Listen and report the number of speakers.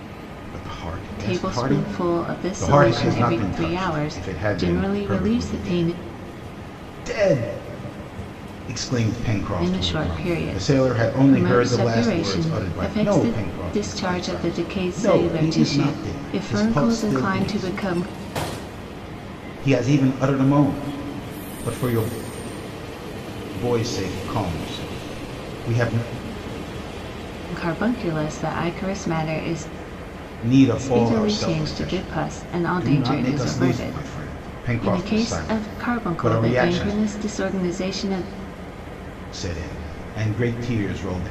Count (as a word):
two